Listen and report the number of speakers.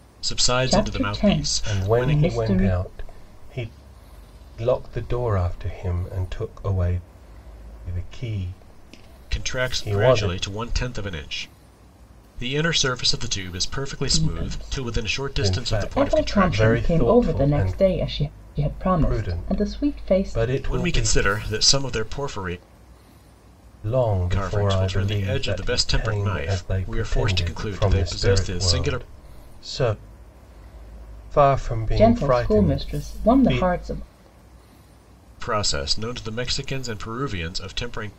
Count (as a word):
three